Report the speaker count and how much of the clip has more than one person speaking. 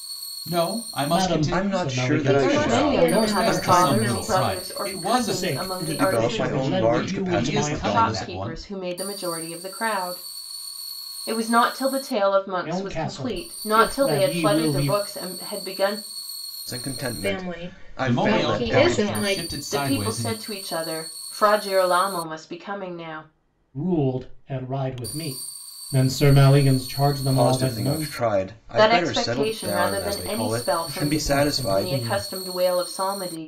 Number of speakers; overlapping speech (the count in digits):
5, about 53%